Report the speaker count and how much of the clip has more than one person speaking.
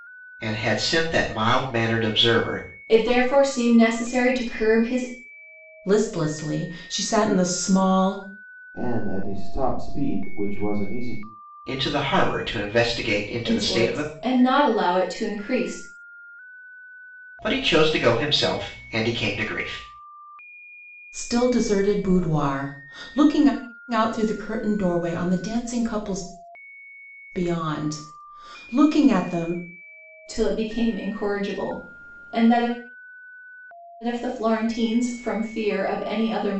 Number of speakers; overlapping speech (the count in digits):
4, about 2%